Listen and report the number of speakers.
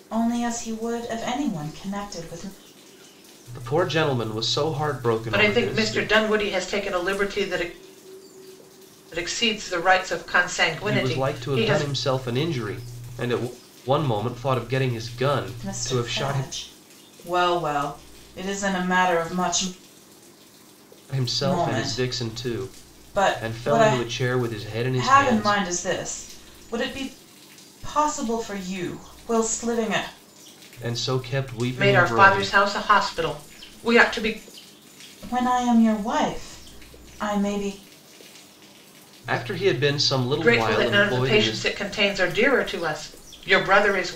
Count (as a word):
three